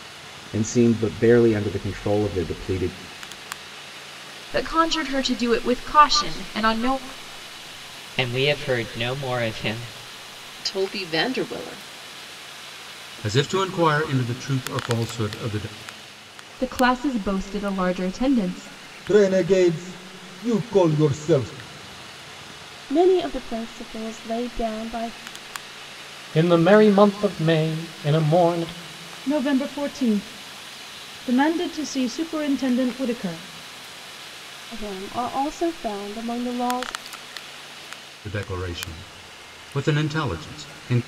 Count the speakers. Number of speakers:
10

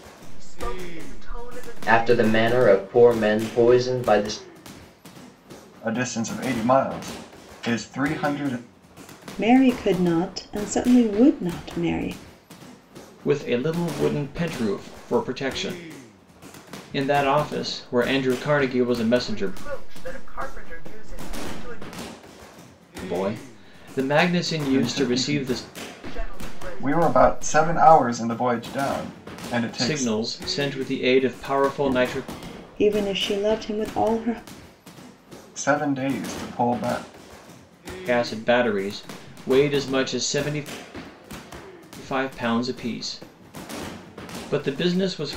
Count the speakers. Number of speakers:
5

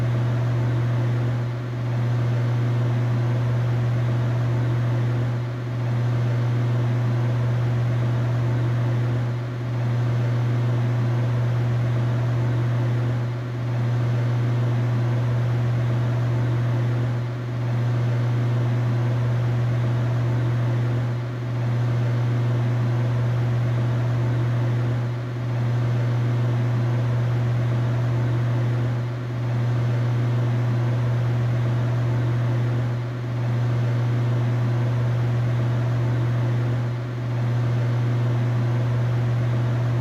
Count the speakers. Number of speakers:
0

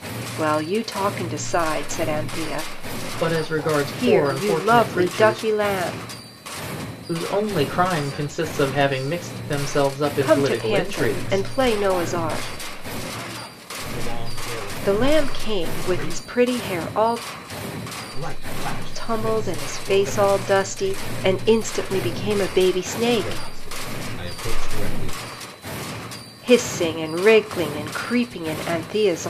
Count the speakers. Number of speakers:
3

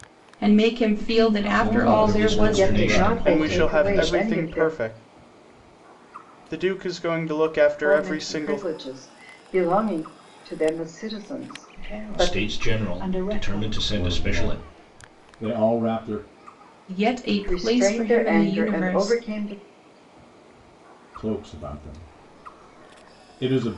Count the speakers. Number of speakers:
6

